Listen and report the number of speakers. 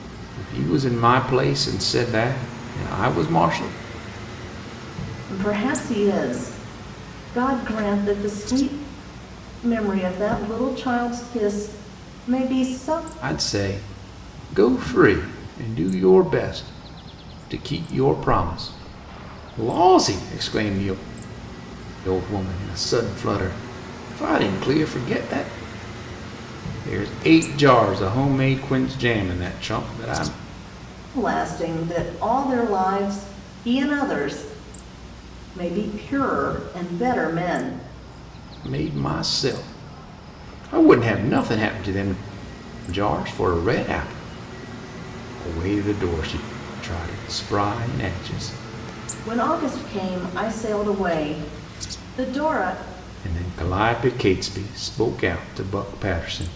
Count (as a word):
two